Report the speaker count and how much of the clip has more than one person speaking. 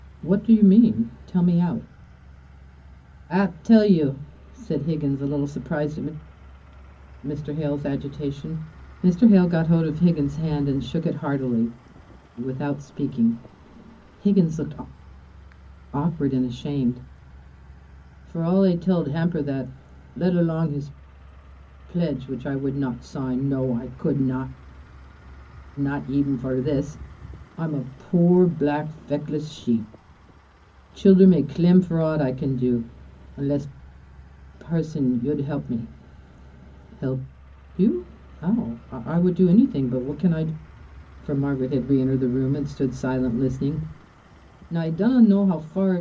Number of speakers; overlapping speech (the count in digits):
1, no overlap